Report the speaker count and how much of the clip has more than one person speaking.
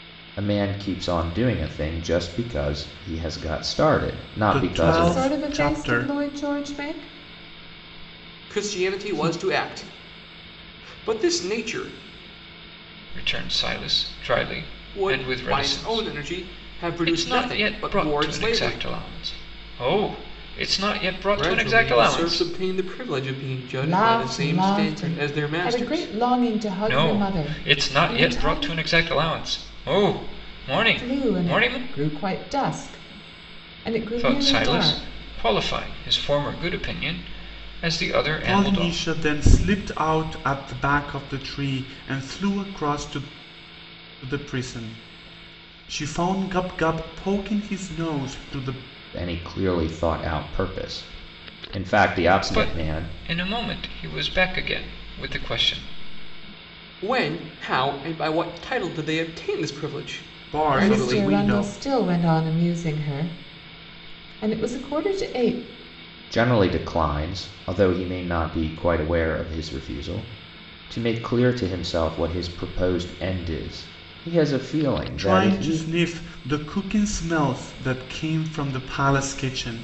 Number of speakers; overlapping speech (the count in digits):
5, about 22%